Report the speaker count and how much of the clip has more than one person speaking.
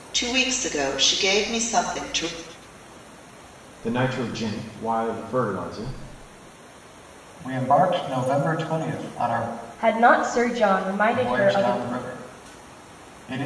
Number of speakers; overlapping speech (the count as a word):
four, about 5%